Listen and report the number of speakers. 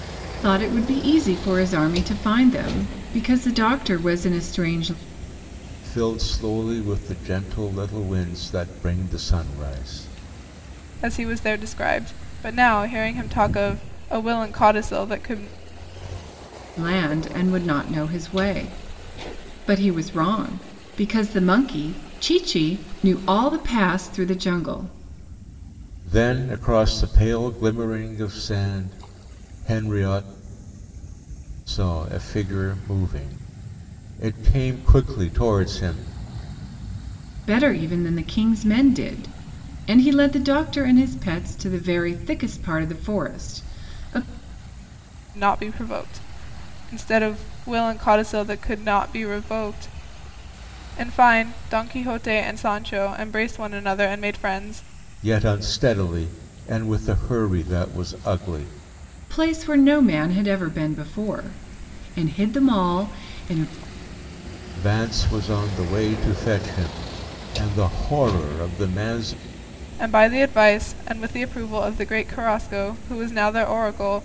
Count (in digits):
3